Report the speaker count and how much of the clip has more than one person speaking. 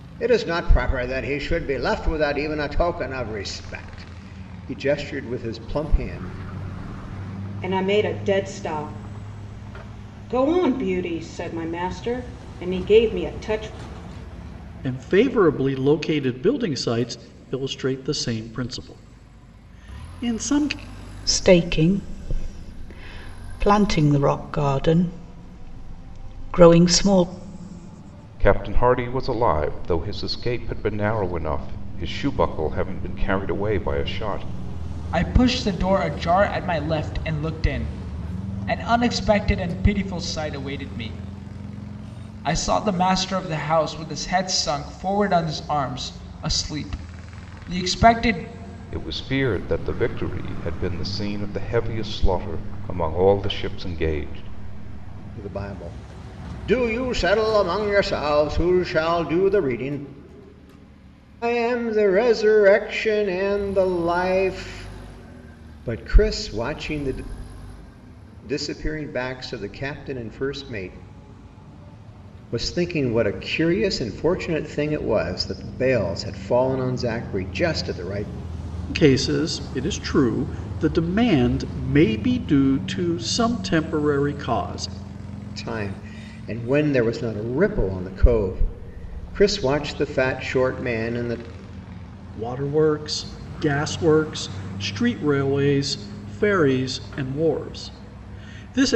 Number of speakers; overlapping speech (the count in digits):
6, no overlap